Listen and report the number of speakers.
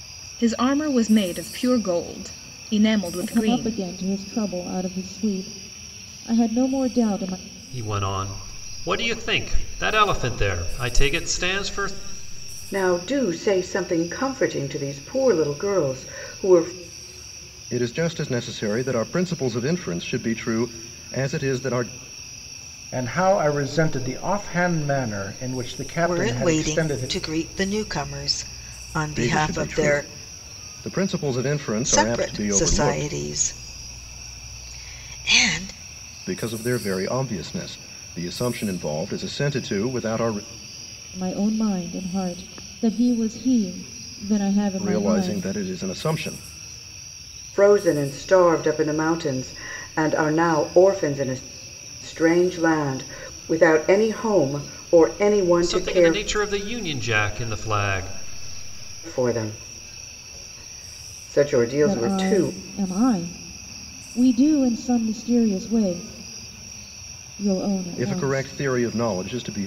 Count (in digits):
7